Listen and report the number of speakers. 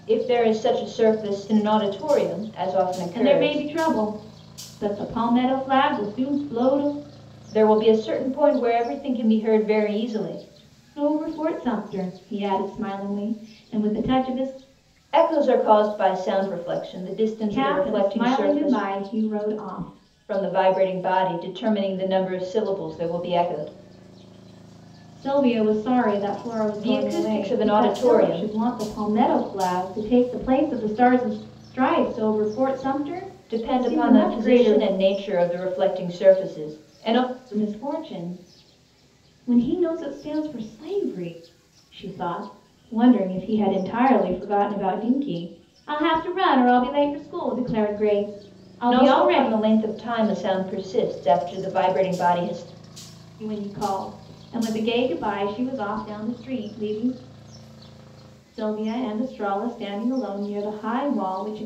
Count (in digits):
2